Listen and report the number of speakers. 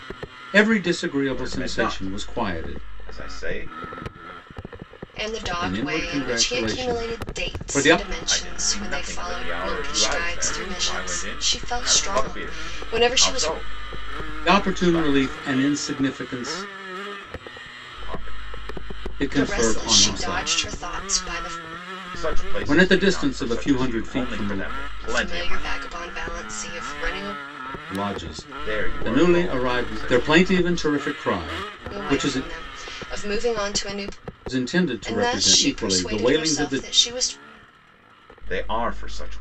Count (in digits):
3